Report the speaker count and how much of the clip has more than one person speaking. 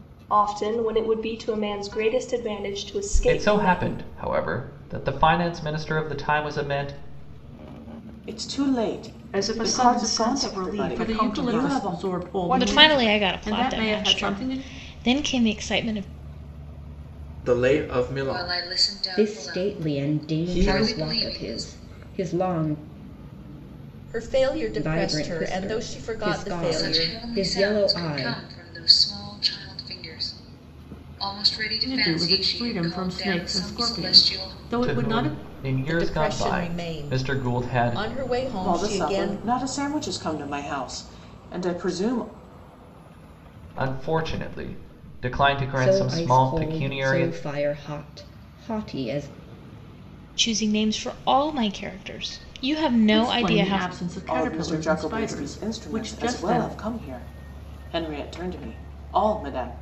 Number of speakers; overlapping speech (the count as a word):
ten, about 40%